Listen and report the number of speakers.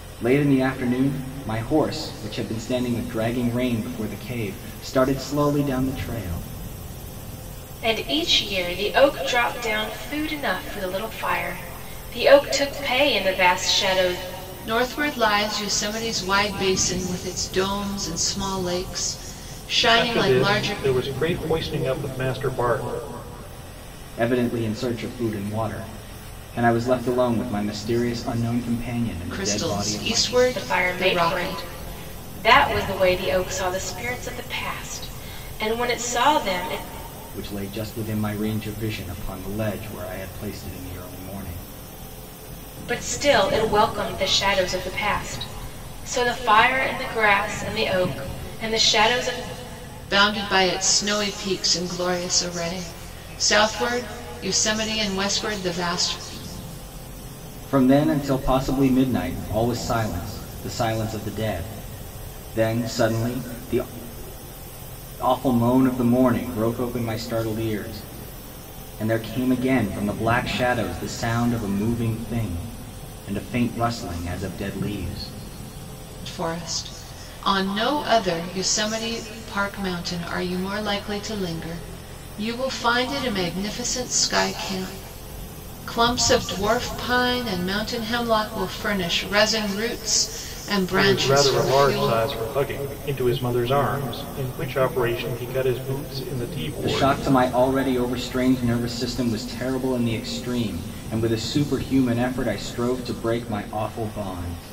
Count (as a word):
four